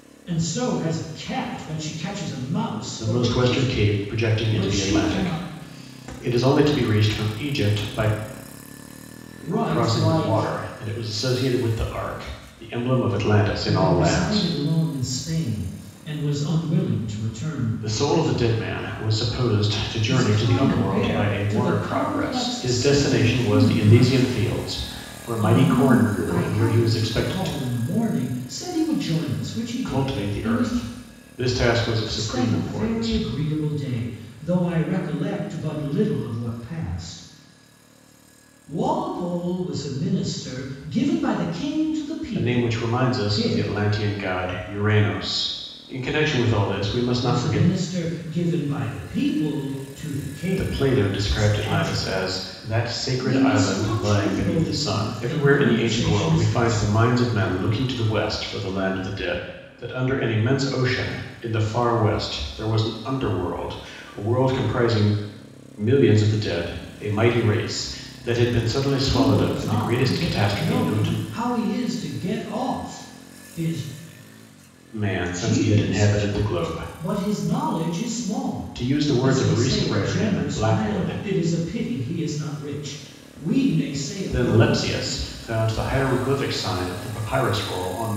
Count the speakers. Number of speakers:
2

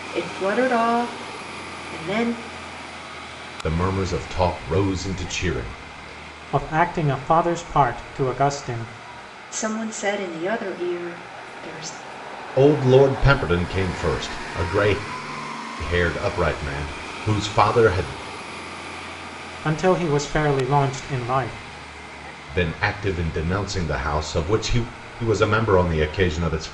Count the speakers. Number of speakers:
3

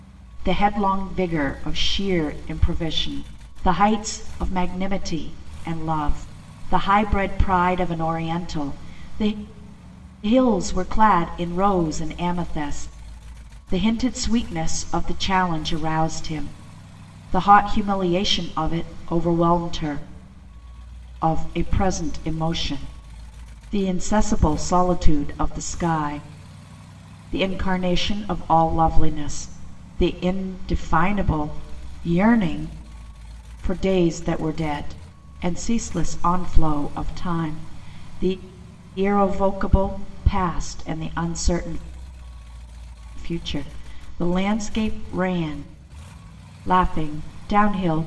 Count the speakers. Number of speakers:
1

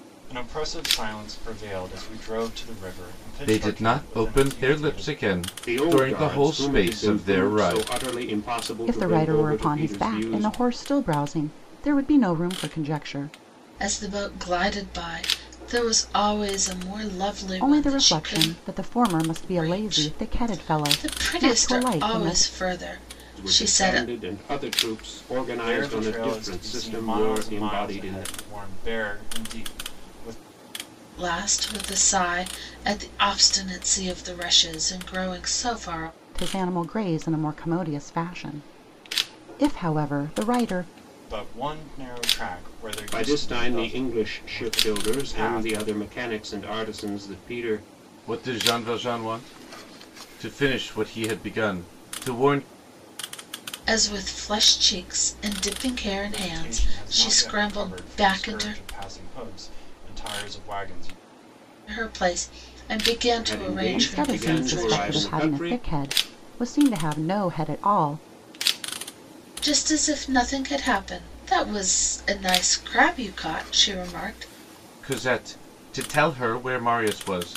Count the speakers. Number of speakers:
5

